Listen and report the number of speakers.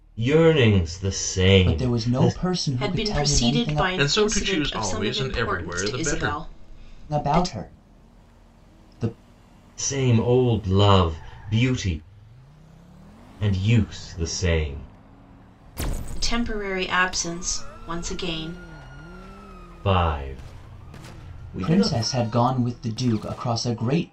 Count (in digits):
4